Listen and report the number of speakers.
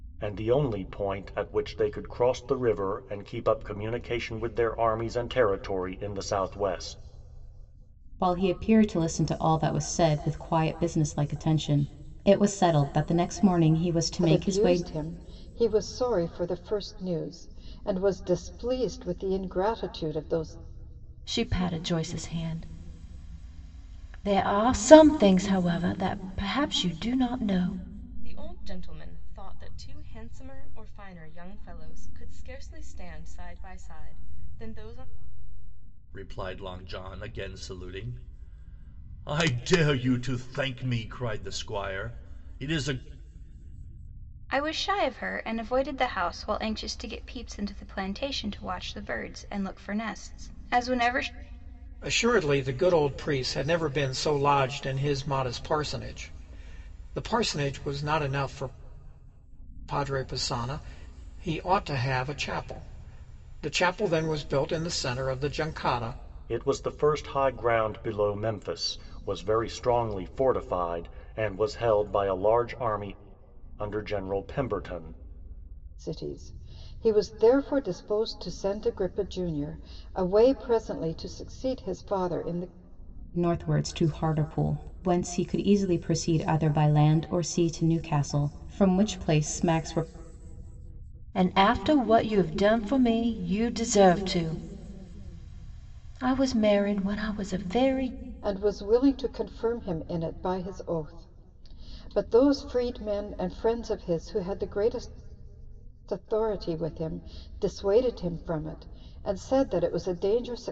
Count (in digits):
8